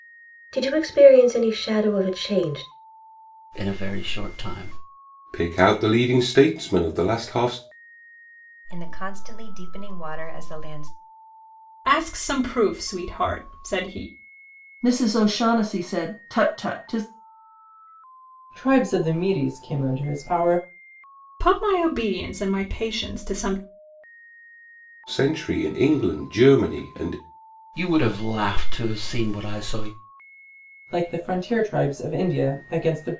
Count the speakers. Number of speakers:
seven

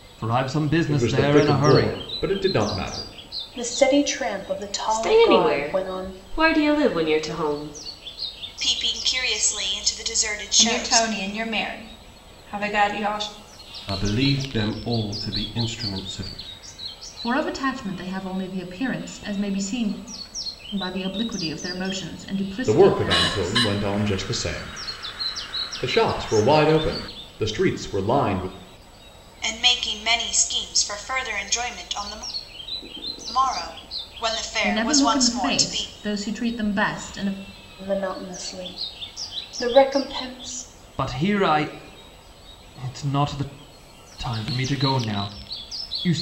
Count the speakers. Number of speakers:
eight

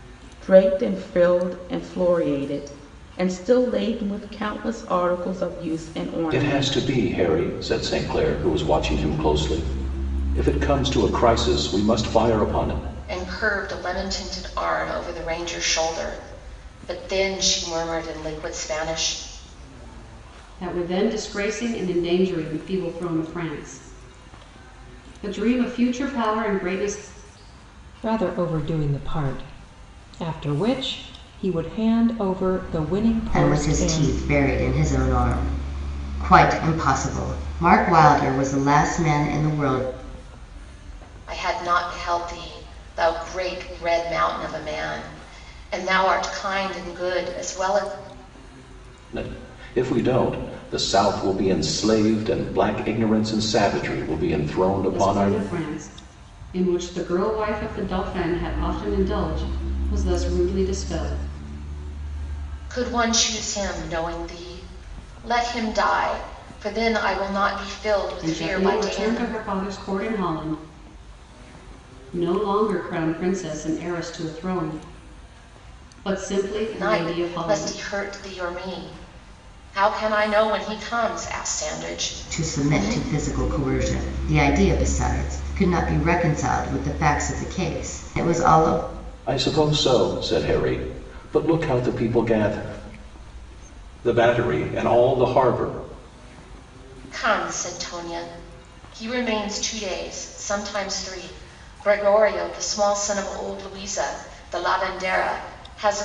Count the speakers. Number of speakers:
six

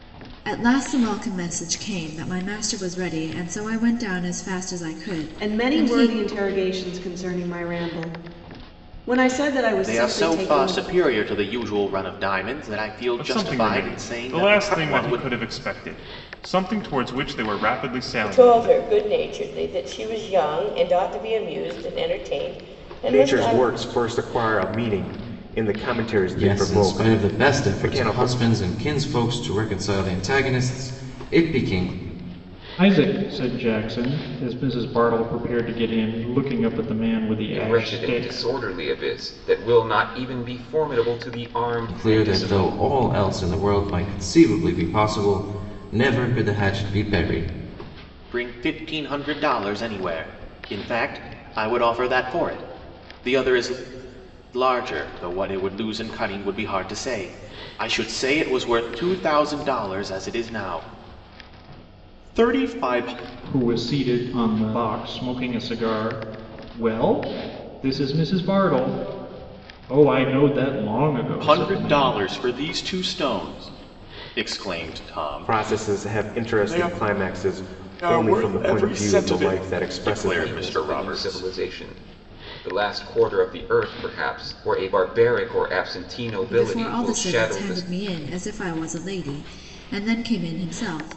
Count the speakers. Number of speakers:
nine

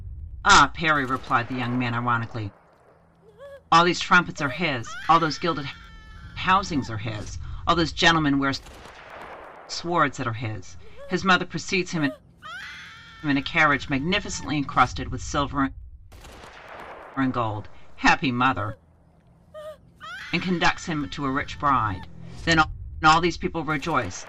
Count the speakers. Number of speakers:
one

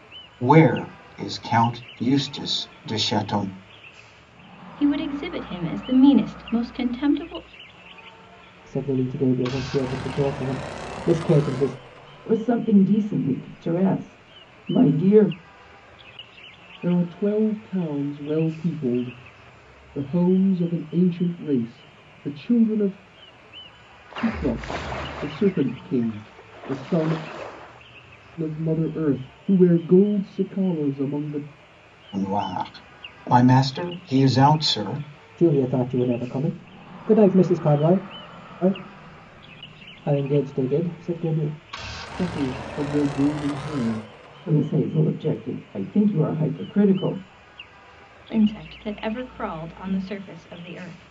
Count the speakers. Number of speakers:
five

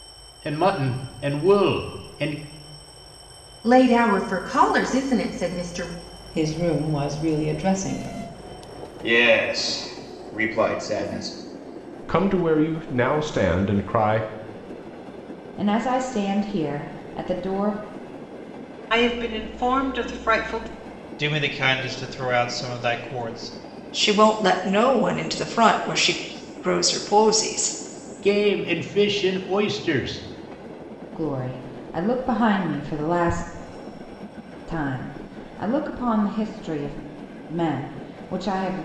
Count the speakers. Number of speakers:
nine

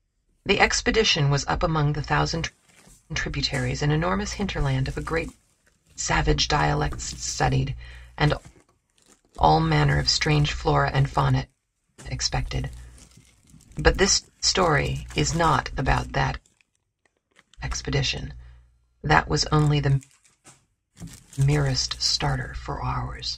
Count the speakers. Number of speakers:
one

